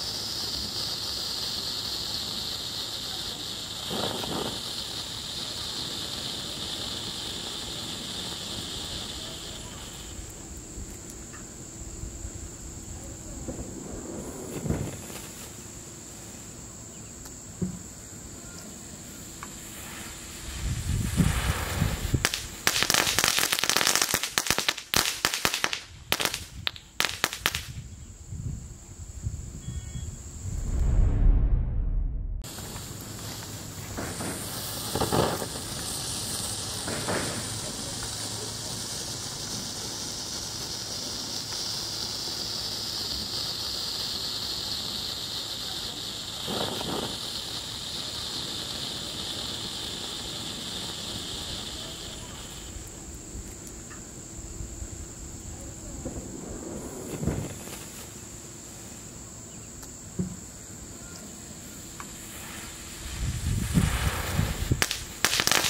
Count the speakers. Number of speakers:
zero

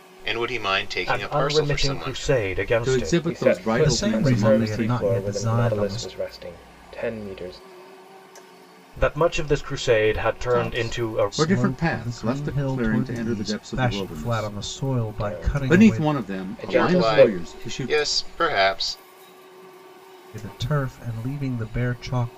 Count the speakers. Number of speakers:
five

